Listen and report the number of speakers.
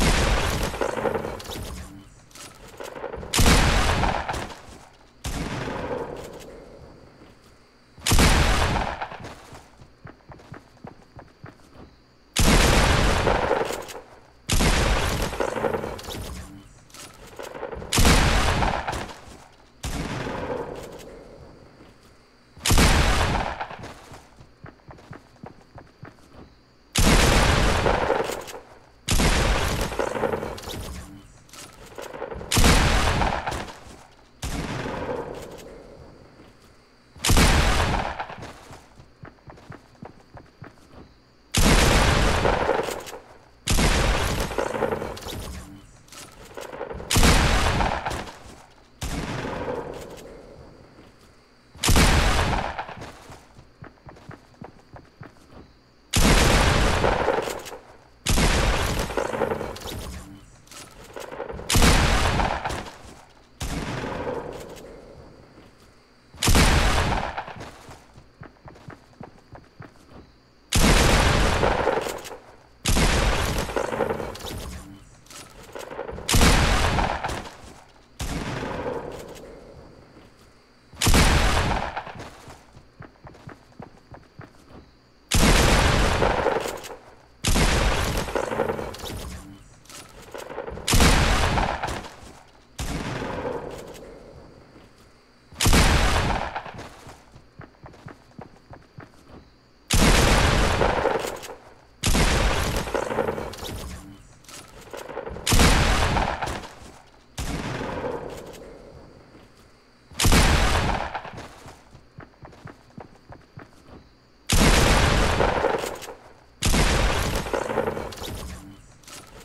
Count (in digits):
0